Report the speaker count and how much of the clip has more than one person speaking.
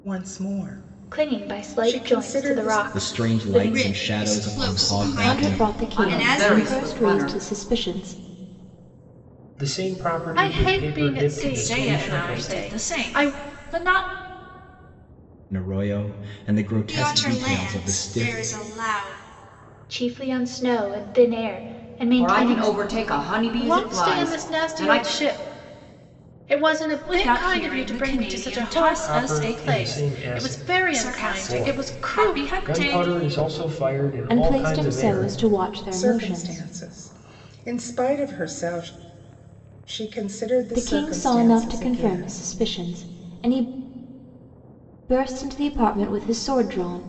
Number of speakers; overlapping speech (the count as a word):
nine, about 48%